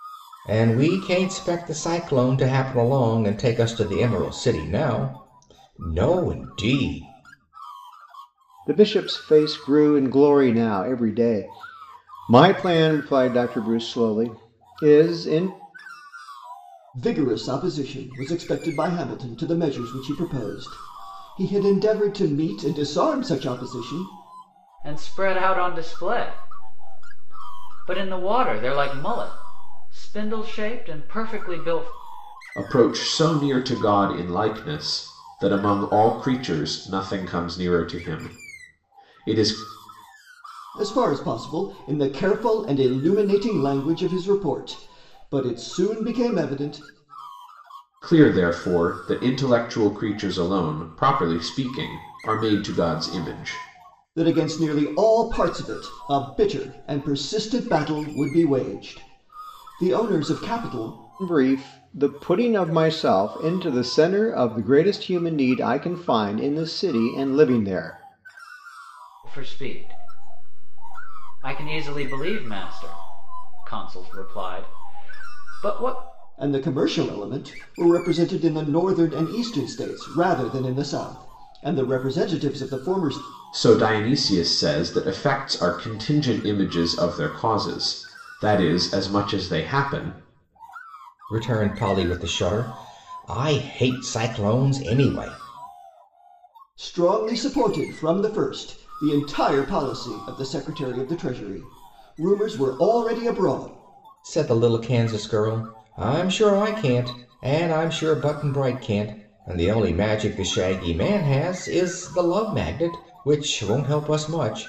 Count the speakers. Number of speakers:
5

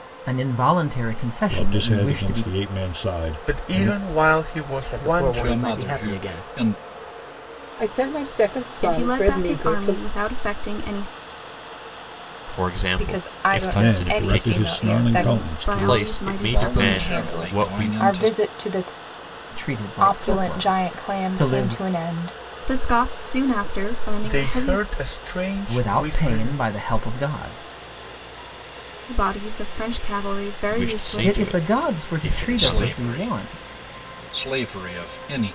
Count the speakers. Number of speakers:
9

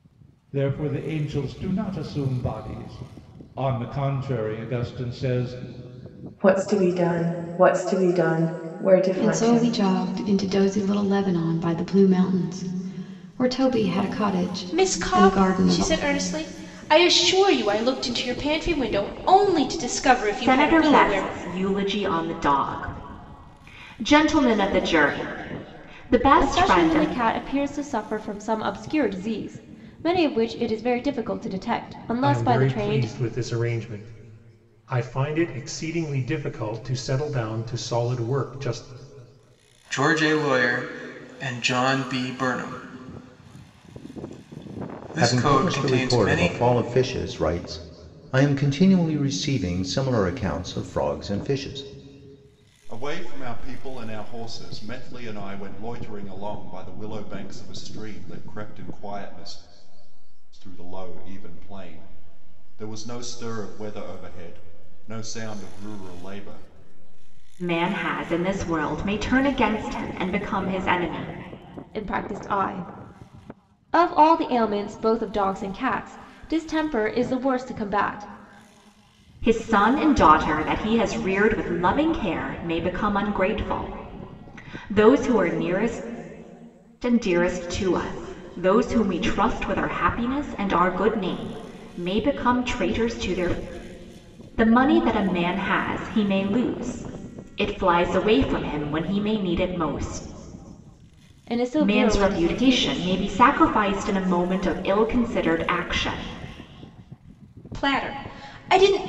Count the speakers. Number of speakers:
10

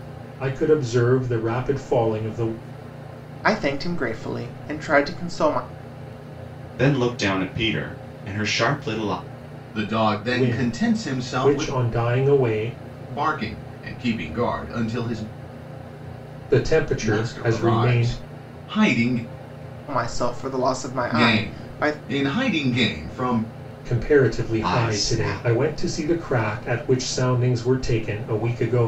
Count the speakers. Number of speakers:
4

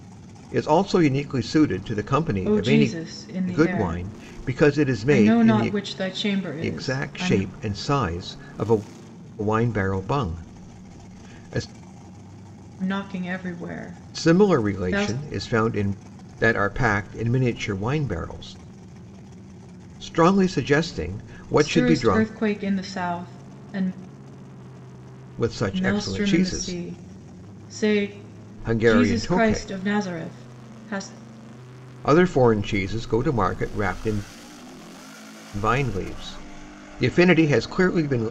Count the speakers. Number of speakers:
2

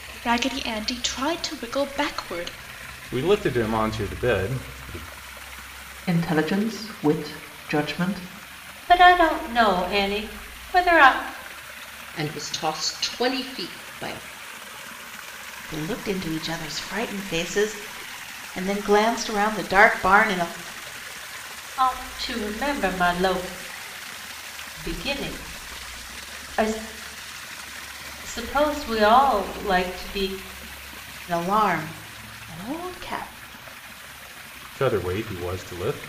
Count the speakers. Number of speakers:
6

